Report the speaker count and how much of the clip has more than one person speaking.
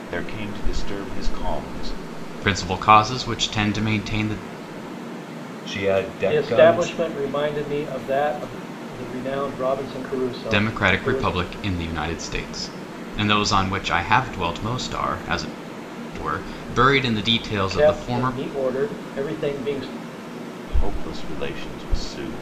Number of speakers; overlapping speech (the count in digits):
4, about 11%